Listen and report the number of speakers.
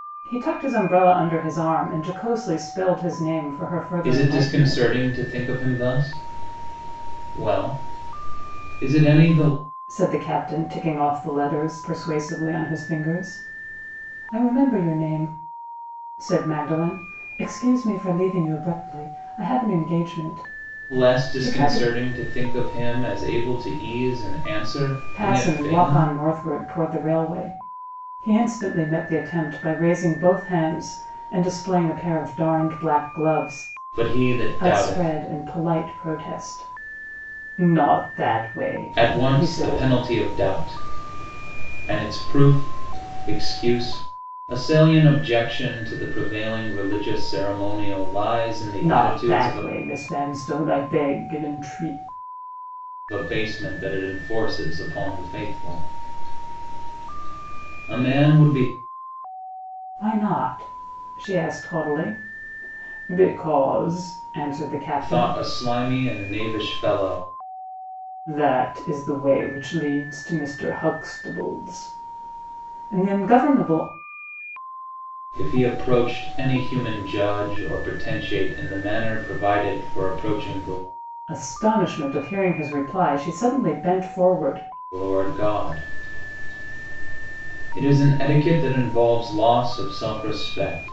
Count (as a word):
two